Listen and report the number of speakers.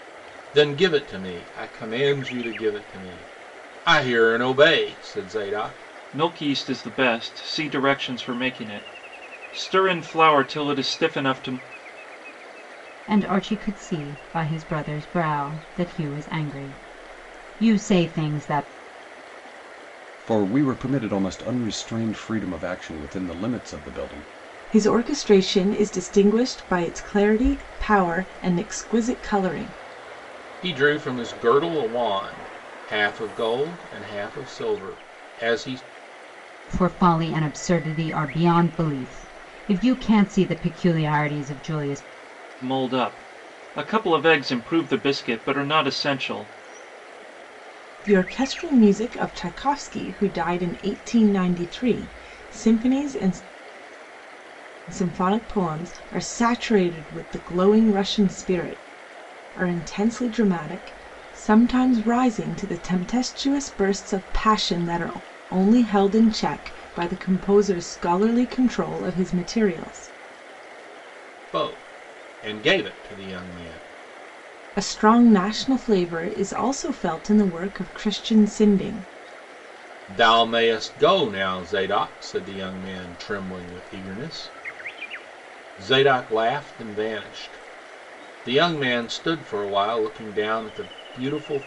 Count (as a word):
five